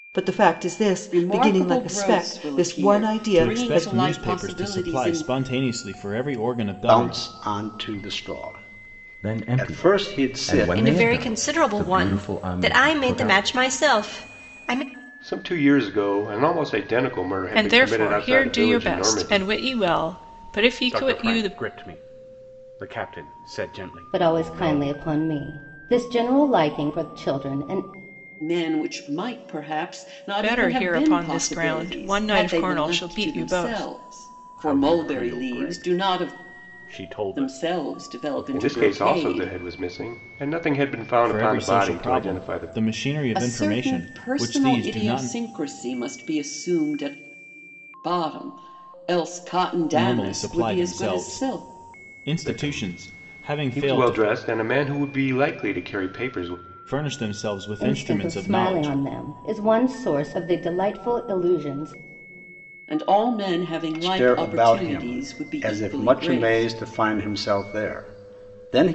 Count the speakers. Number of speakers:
10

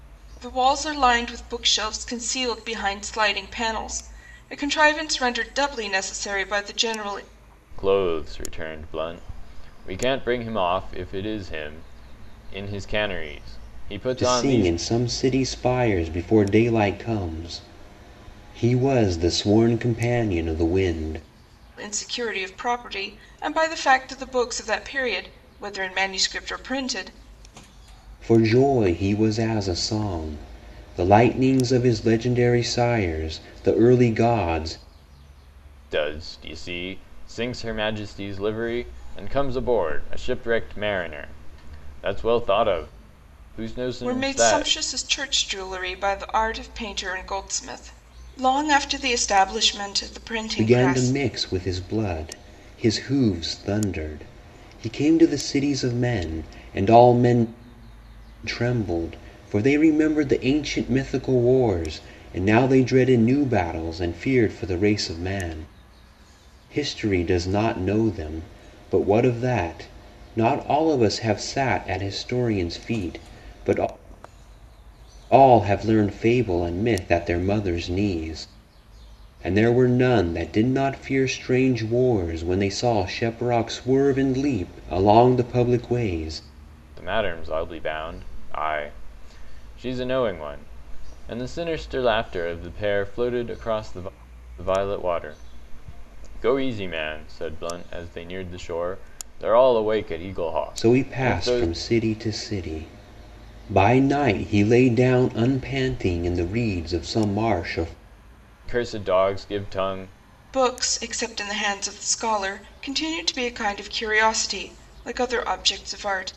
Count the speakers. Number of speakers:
3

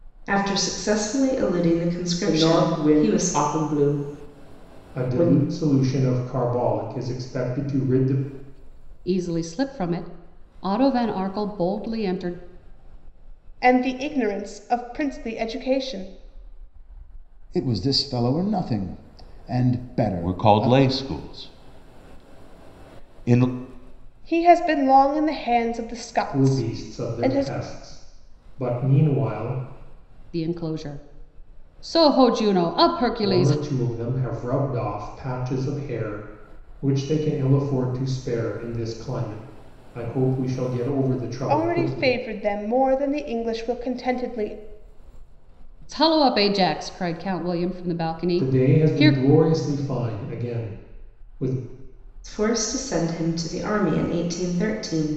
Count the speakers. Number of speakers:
7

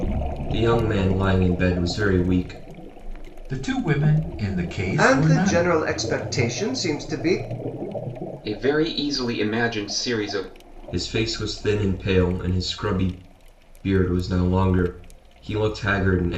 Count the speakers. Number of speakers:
4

